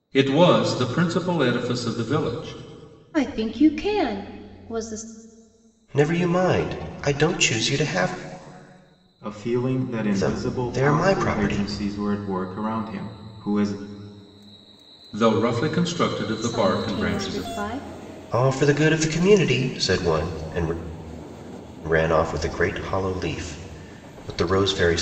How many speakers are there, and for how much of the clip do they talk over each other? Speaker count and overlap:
four, about 11%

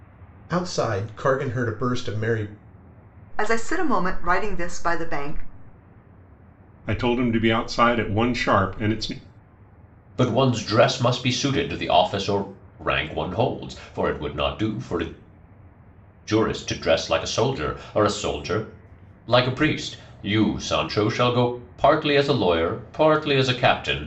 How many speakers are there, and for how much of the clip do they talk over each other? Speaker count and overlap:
four, no overlap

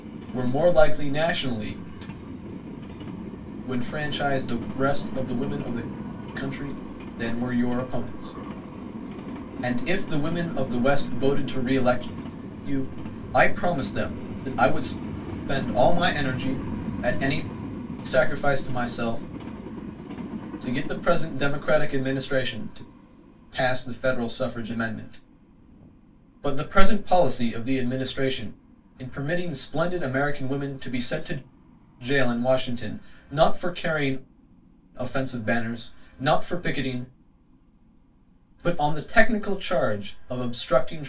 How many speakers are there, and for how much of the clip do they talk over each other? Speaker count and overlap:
one, no overlap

